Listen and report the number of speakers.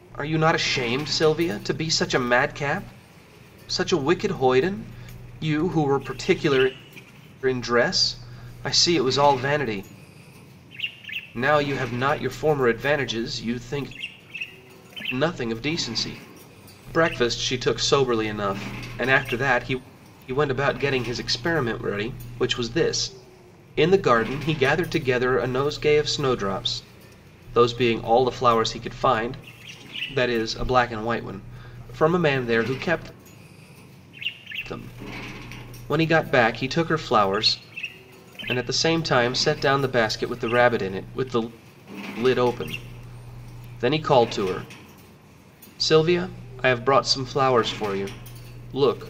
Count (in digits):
1